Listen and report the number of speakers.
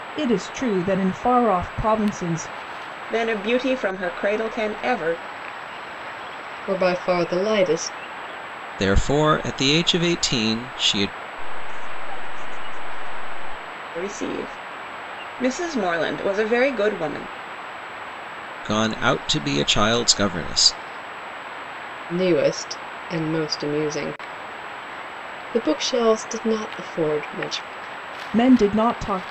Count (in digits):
5